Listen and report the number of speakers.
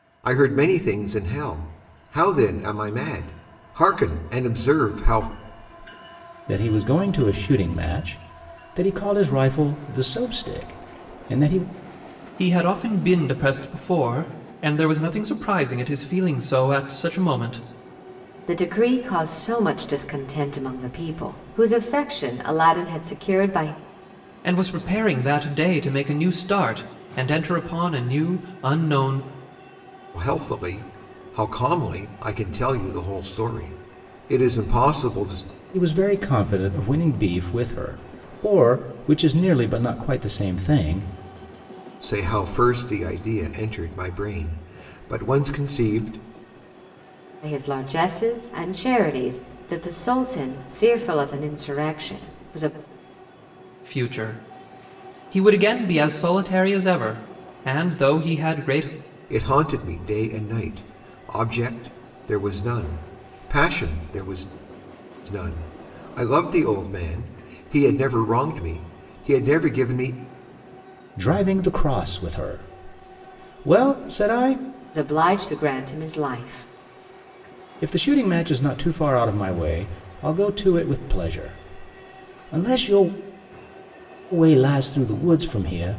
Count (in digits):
4